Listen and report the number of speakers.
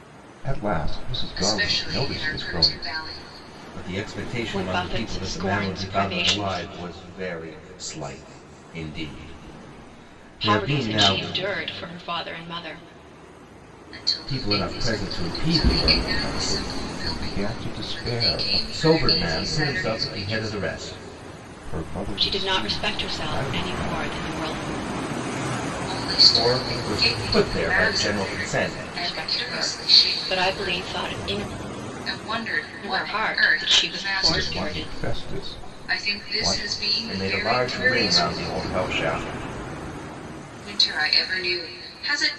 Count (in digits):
4